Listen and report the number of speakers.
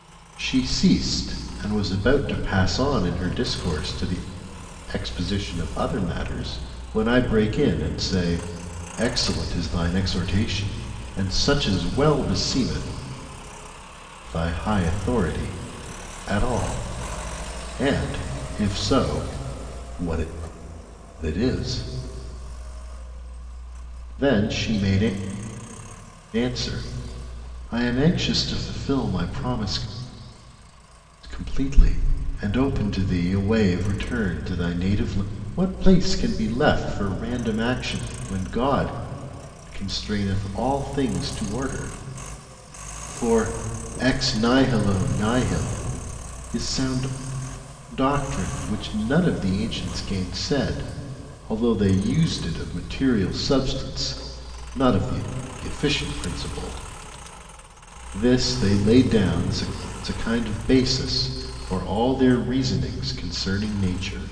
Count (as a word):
one